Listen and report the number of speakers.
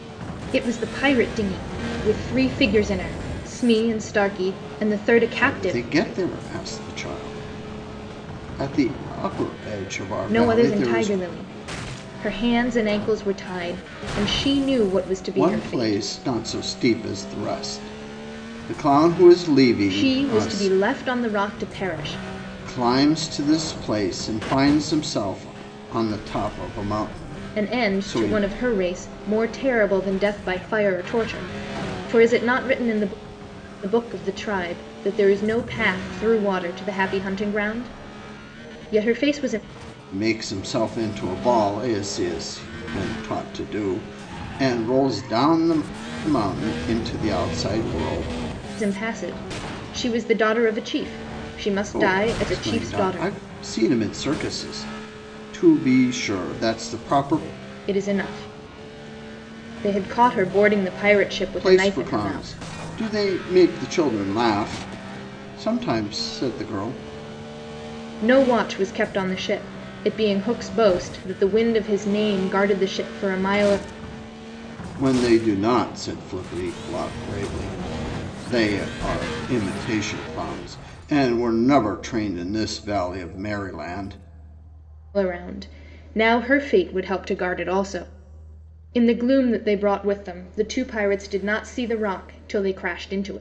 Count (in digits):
2